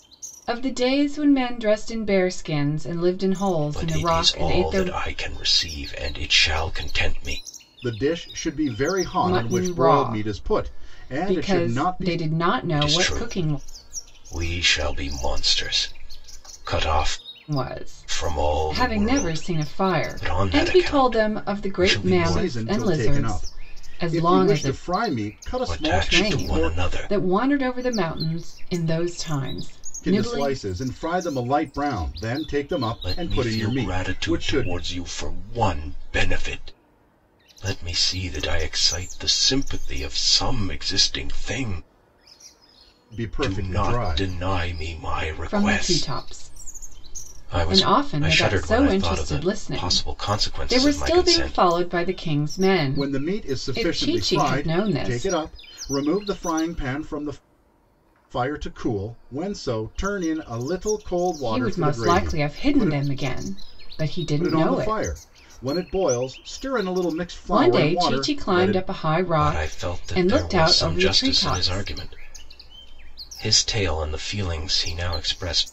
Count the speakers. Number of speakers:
3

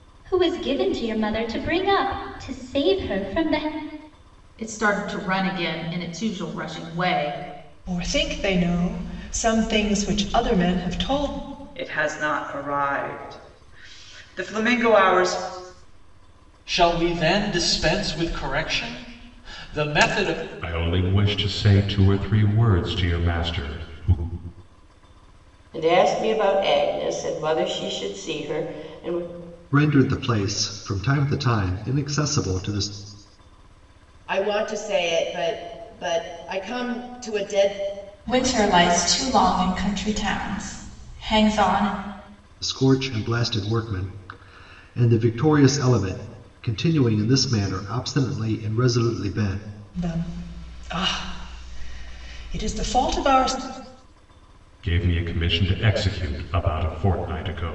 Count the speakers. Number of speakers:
10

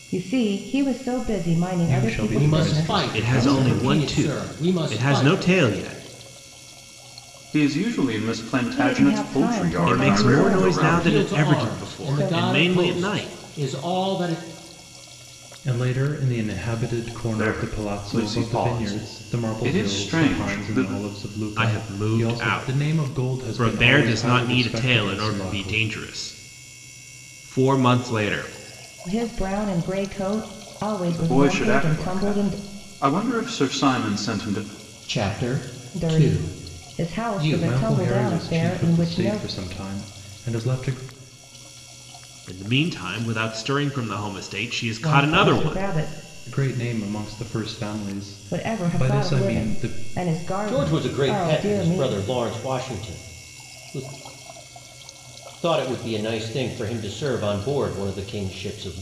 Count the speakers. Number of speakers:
5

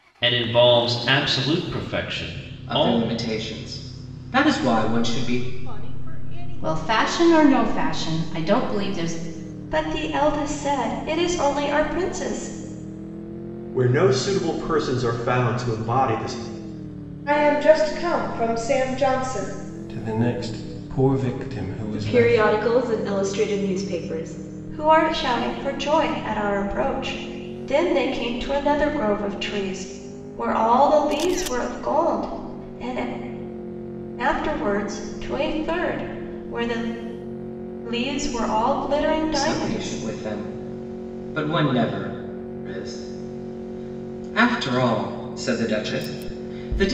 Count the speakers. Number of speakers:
9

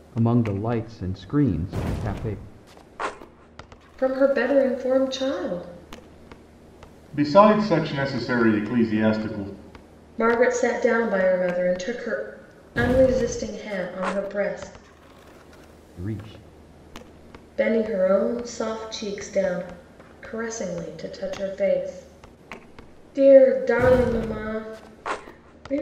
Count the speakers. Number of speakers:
3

